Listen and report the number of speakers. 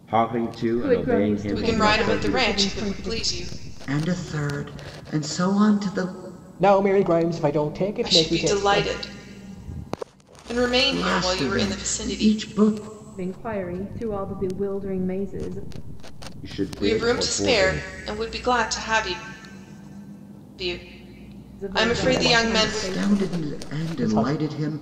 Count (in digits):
5